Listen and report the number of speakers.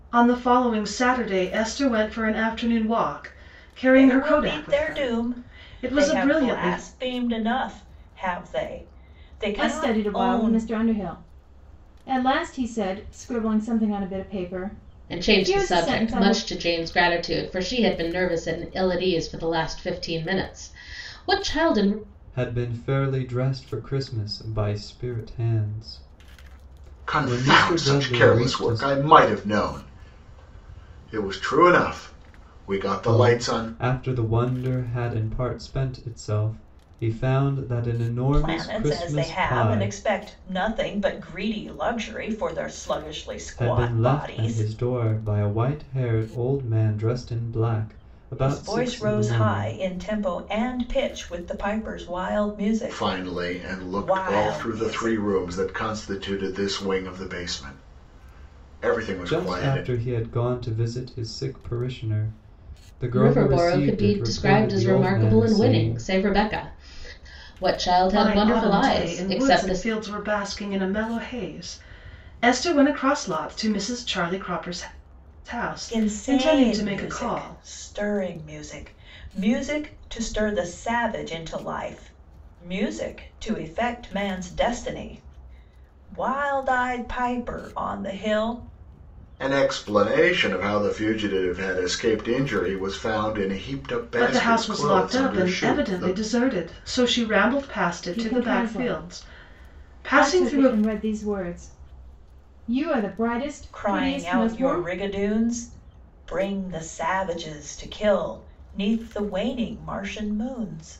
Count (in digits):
6